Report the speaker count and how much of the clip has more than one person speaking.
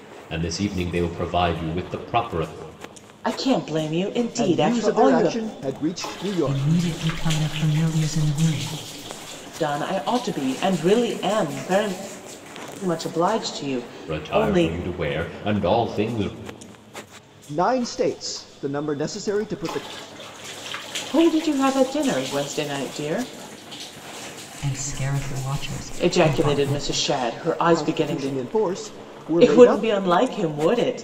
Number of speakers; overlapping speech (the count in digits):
4, about 14%